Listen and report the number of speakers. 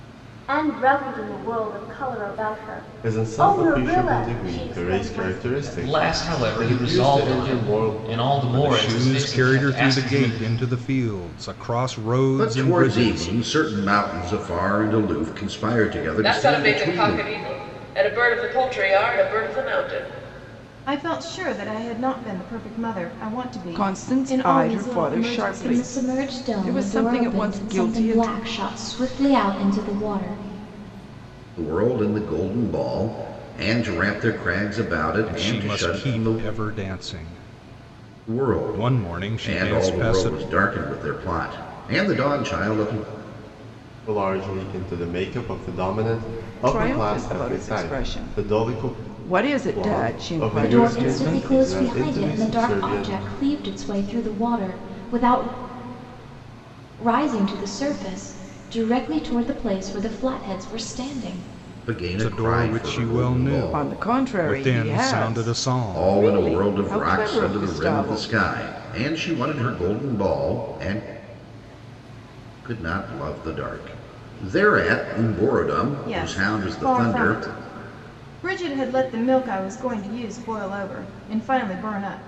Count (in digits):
9